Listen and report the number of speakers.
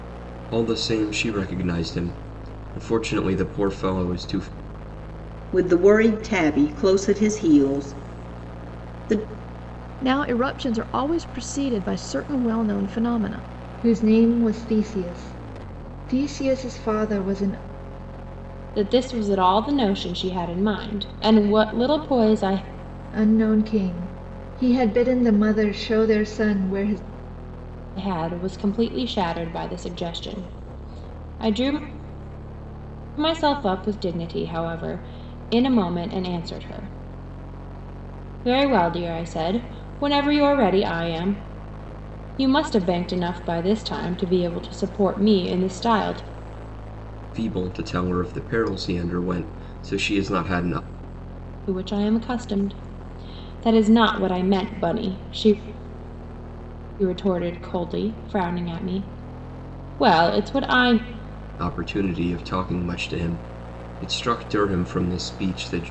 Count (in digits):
5